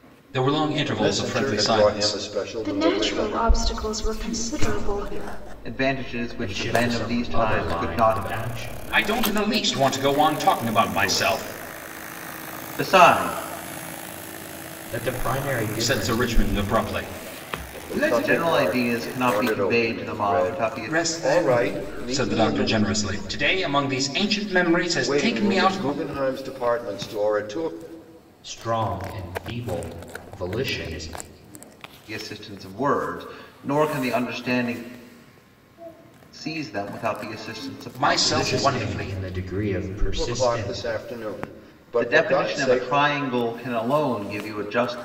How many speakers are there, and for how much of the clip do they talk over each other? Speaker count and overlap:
six, about 41%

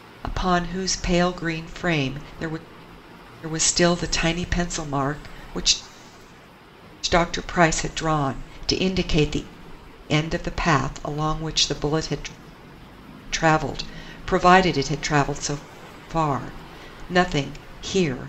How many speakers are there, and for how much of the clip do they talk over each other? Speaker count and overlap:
one, no overlap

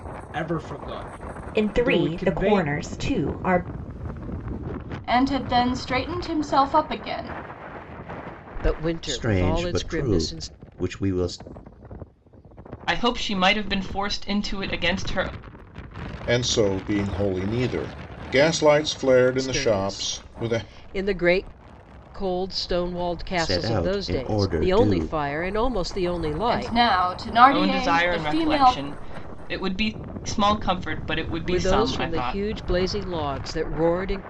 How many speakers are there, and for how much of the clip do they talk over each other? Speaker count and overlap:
seven, about 25%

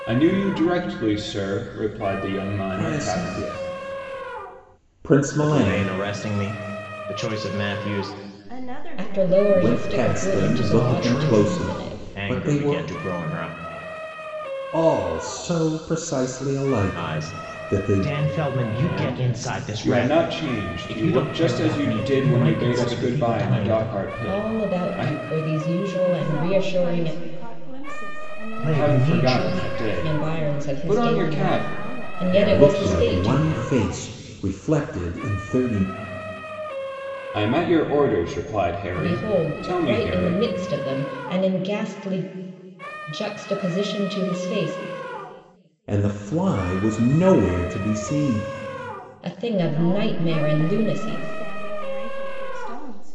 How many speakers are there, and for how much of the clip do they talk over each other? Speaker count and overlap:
five, about 40%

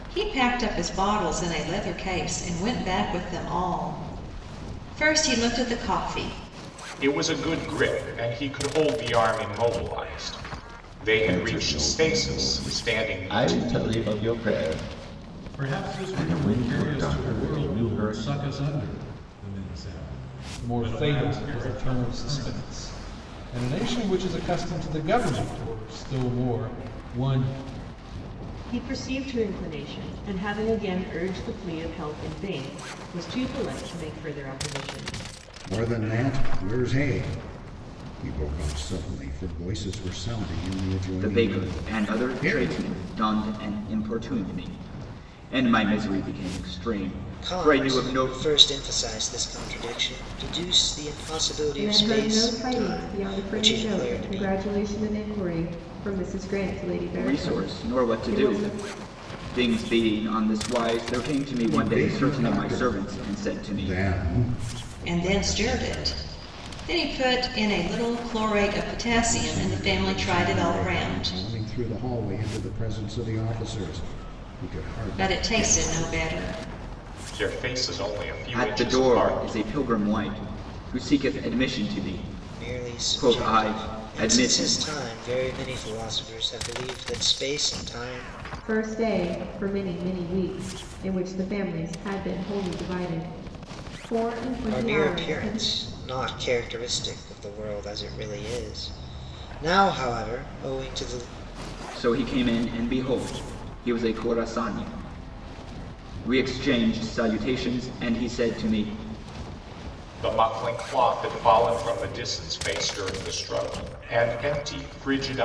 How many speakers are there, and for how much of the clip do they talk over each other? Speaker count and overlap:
ten, about 22%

